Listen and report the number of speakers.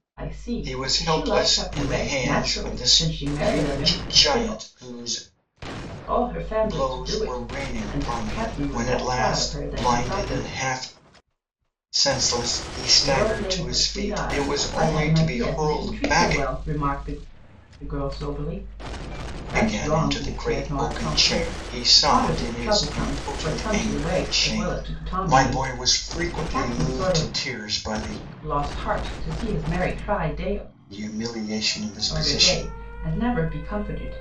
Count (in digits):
2